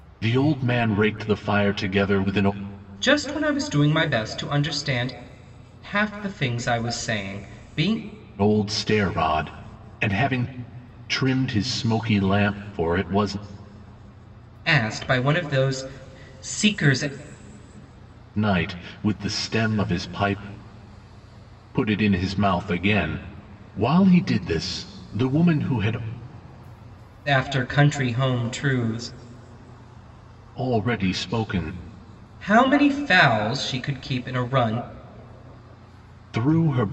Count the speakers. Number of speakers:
2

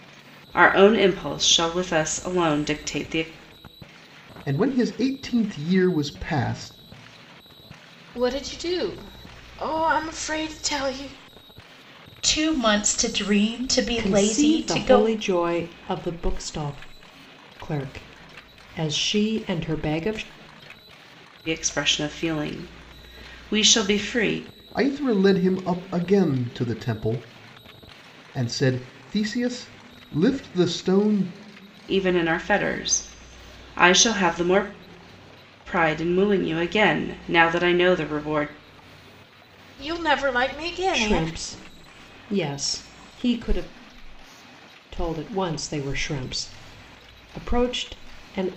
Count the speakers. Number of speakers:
5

